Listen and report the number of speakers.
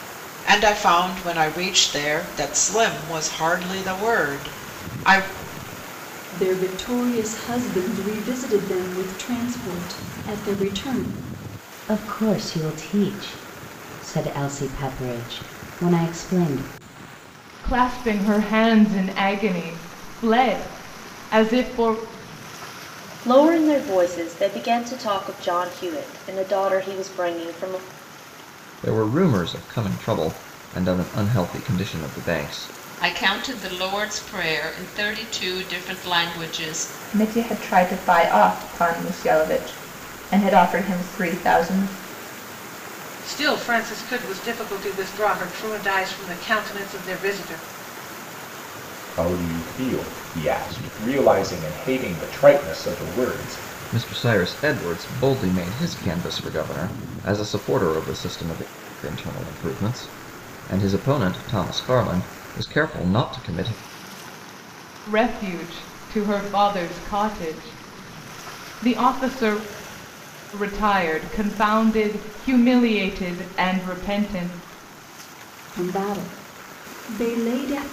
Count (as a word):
ten